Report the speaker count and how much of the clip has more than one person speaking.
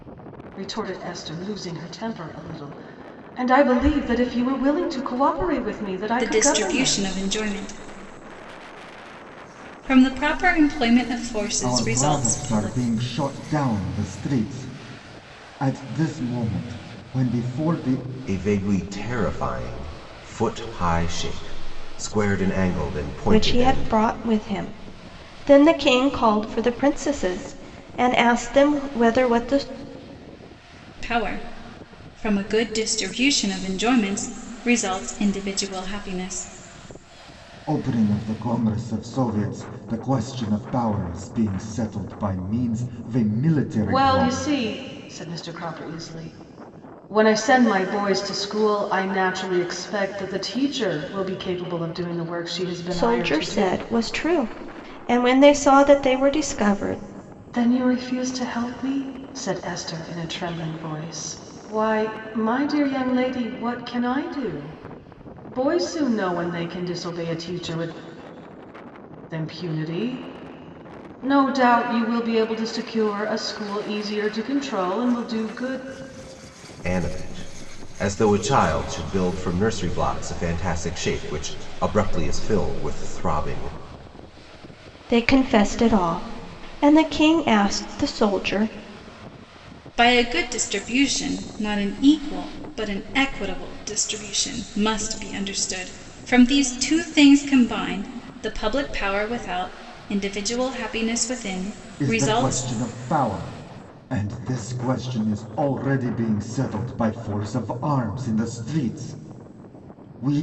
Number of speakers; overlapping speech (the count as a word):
five, about 5%